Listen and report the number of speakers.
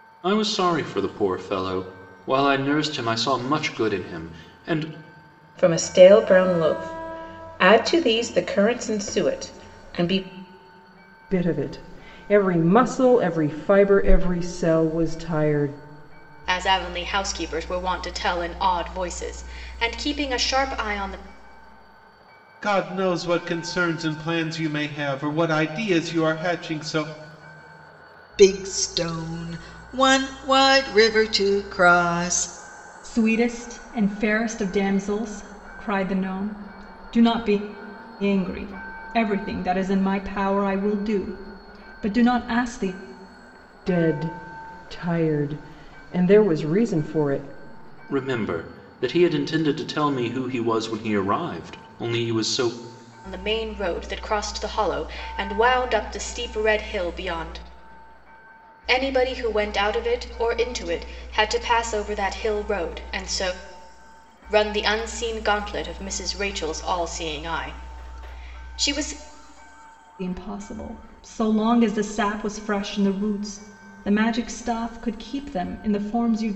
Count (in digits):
7